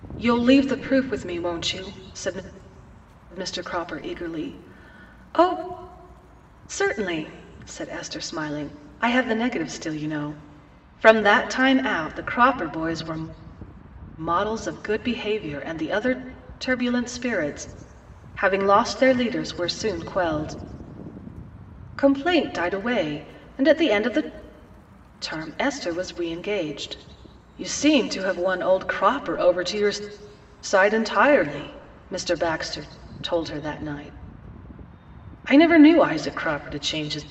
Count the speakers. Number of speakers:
one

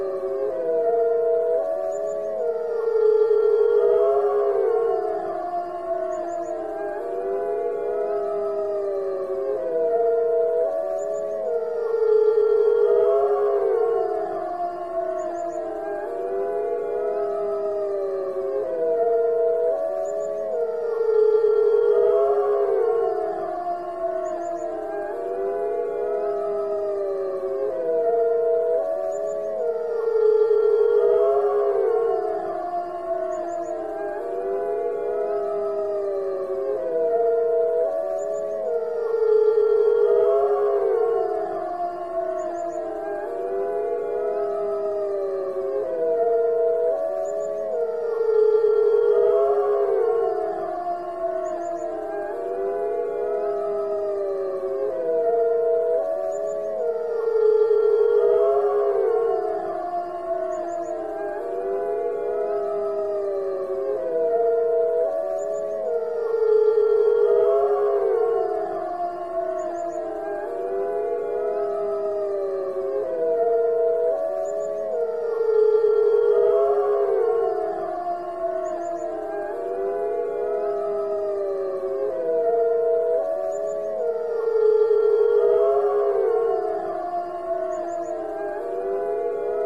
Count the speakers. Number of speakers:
zero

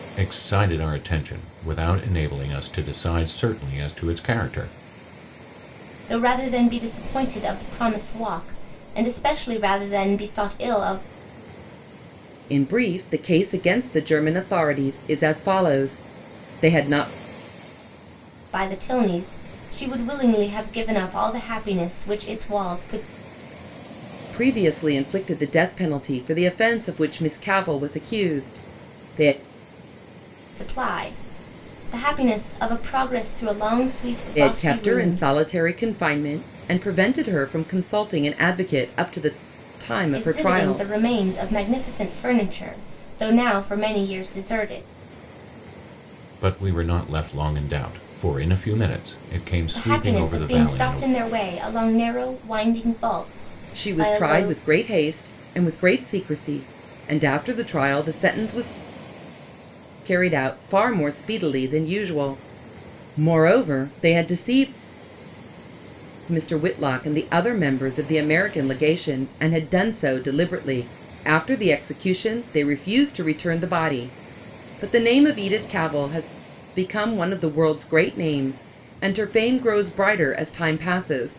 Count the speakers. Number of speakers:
three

